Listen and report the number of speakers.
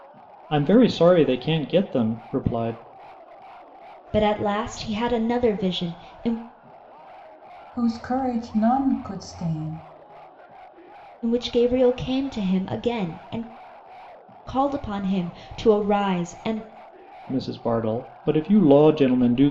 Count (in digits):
3